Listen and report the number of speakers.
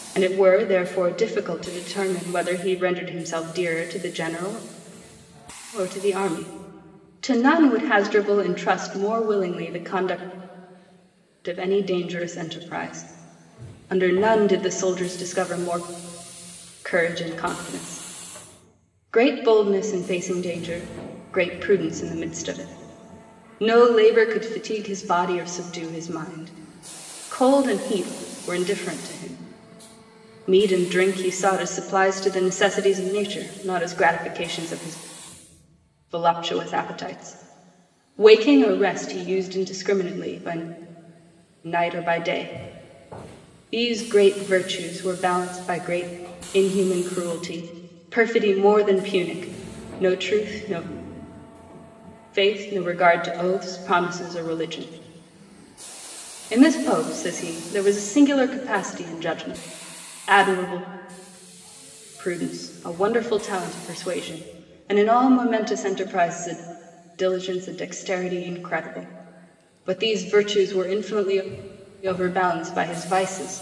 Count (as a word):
one